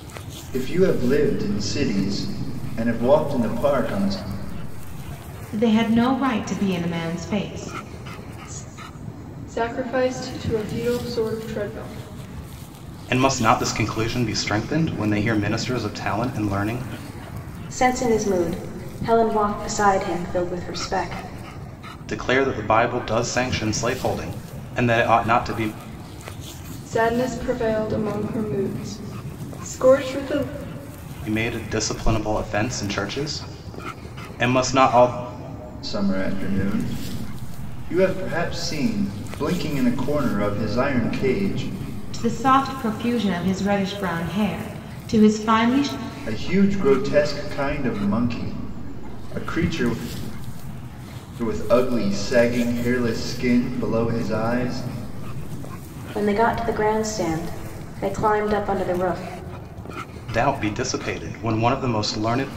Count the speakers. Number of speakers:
5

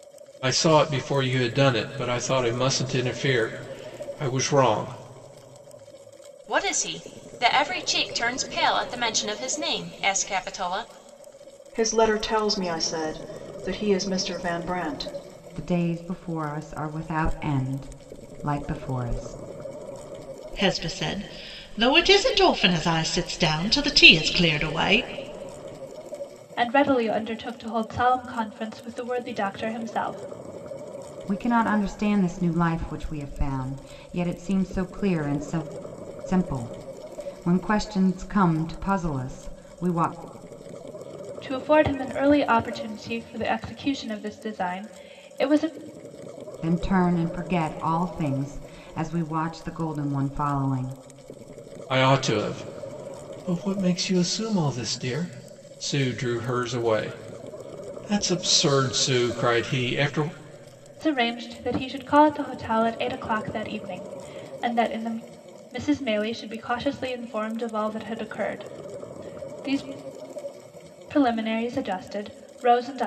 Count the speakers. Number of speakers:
6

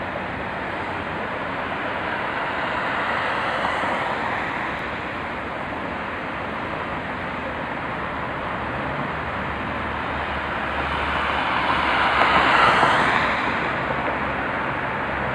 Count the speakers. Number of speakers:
0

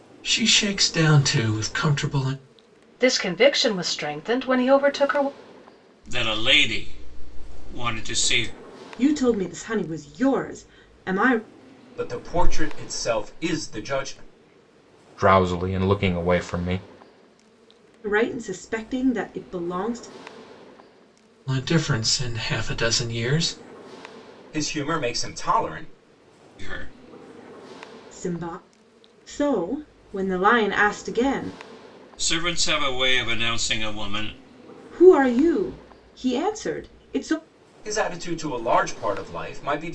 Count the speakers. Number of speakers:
6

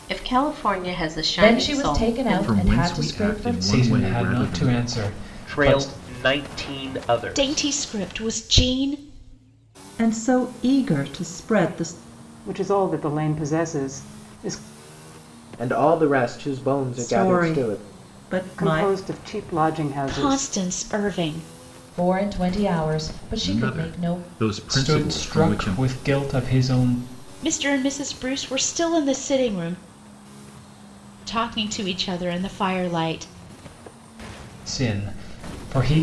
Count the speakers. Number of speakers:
9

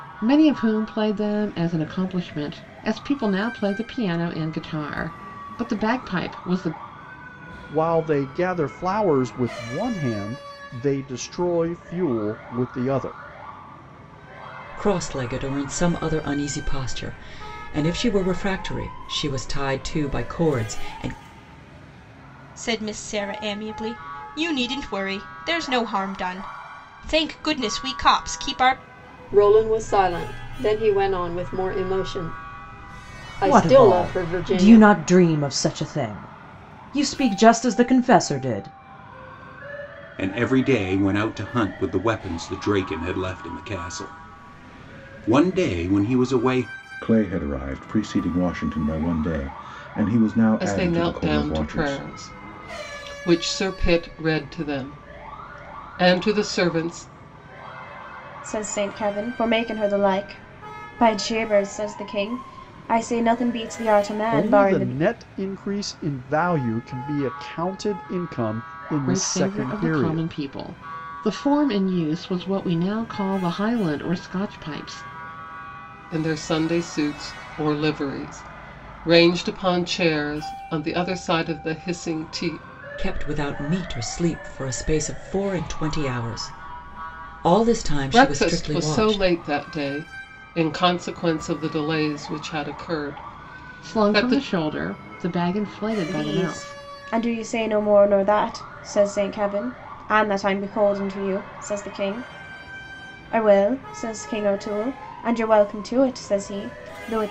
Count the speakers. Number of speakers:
10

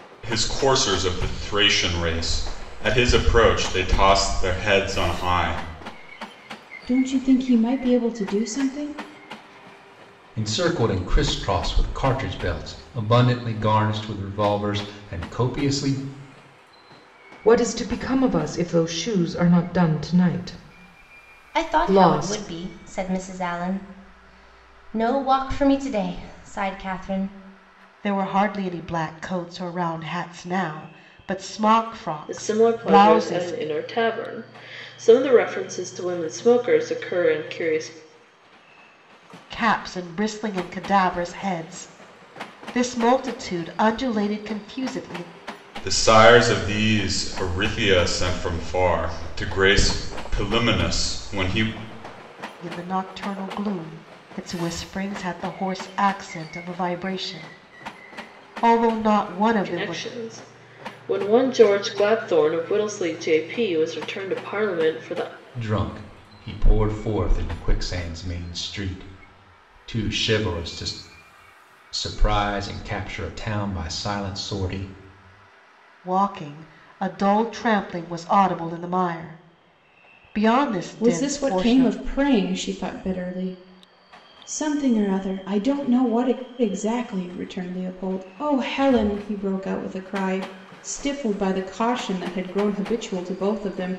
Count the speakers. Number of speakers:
7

